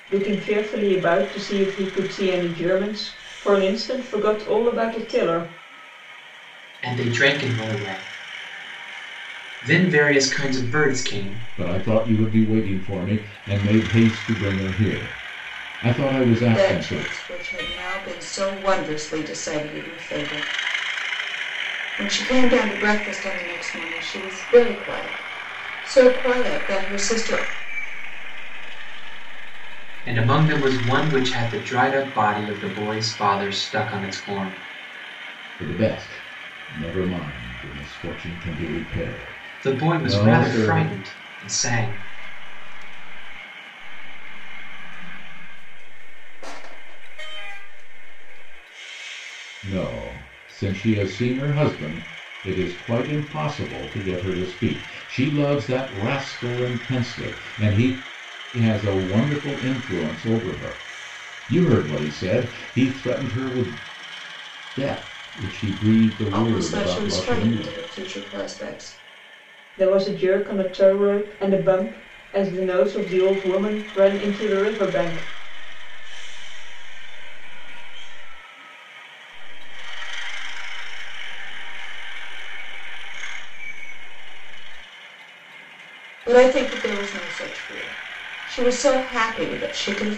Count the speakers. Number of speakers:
five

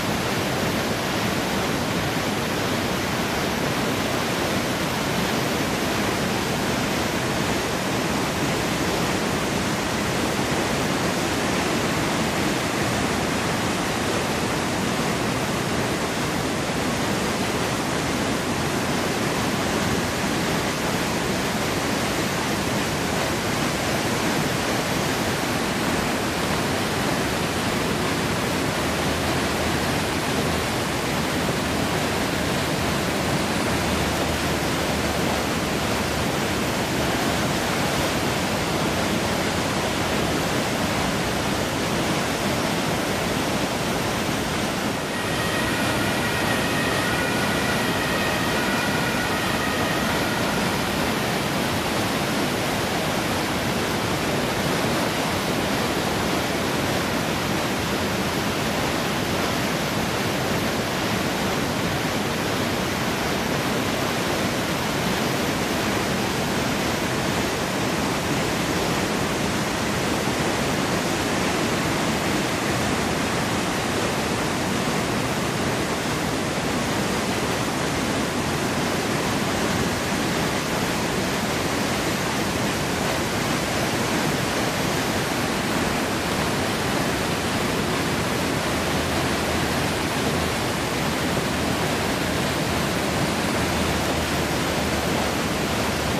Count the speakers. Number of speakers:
zero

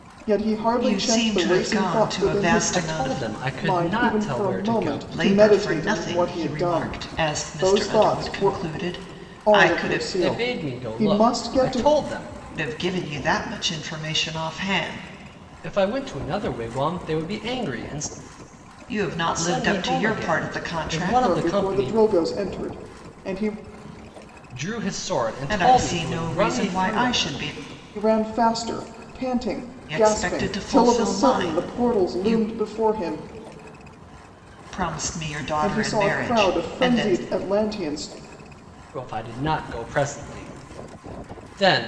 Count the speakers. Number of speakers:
three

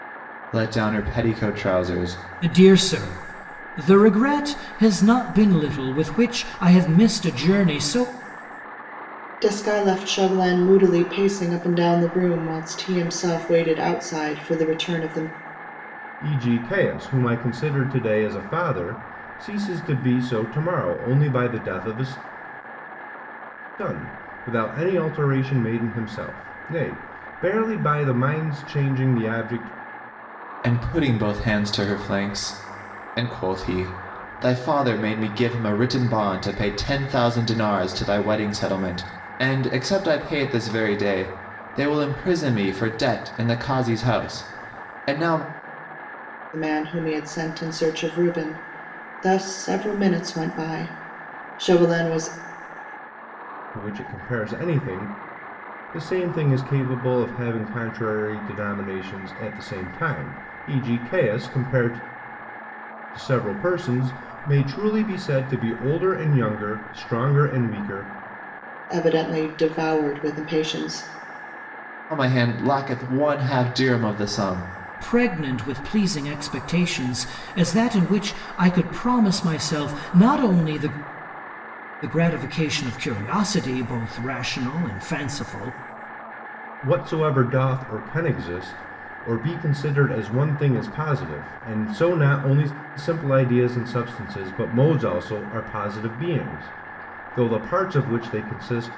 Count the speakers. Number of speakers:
four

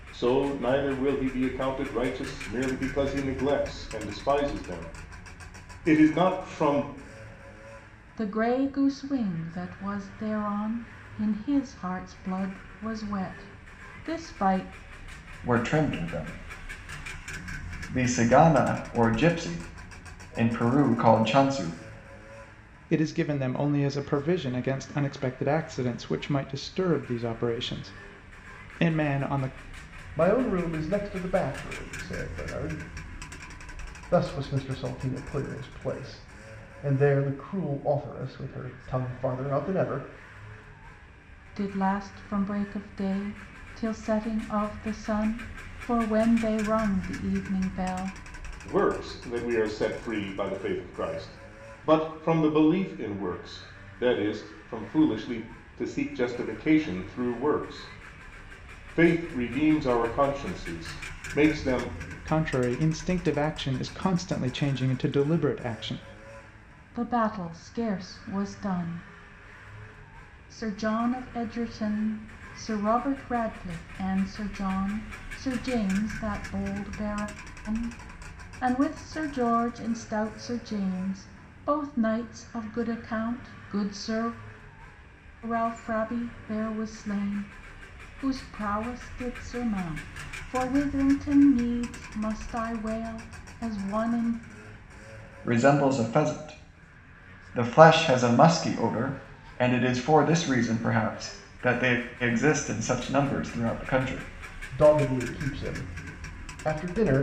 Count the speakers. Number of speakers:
five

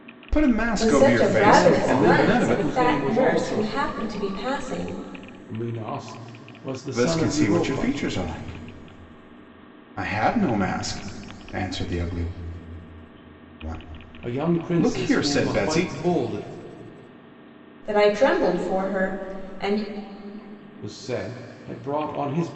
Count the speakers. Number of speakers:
three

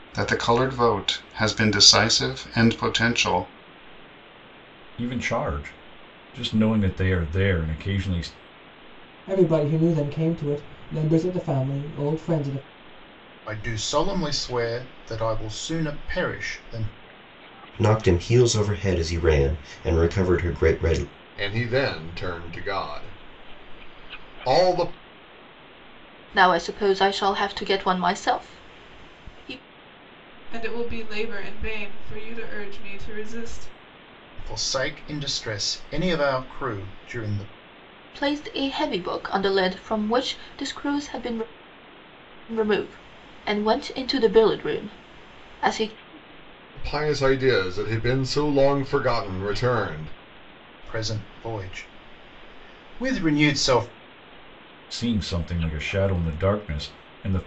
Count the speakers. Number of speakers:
eight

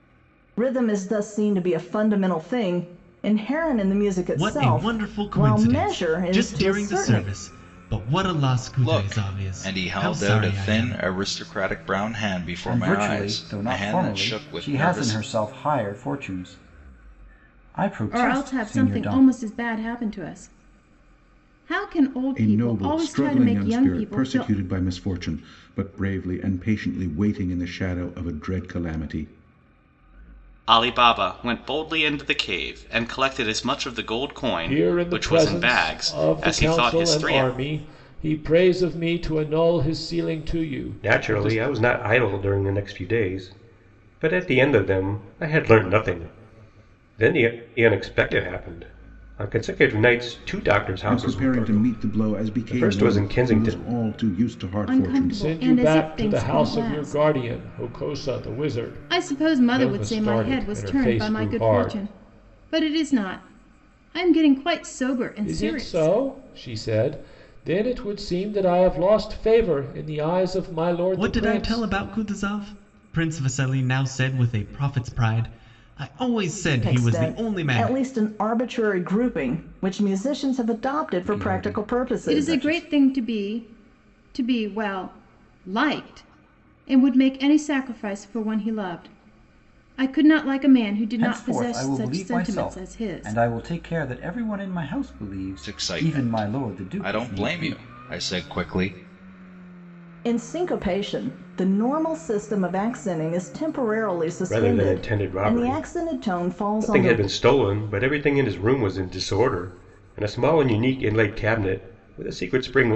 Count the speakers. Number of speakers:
nine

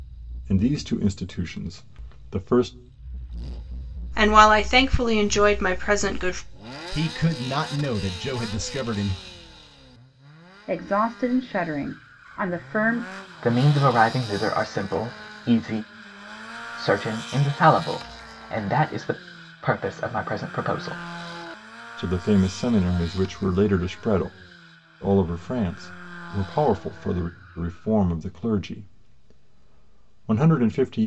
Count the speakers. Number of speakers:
five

